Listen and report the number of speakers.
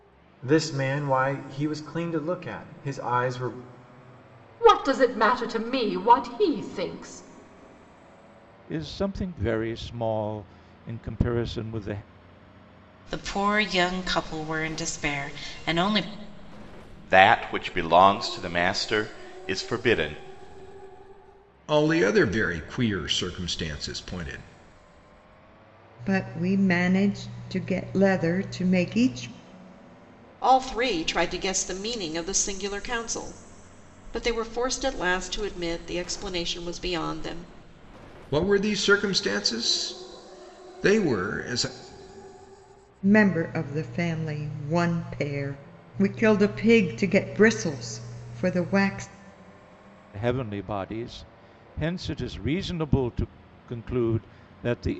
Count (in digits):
8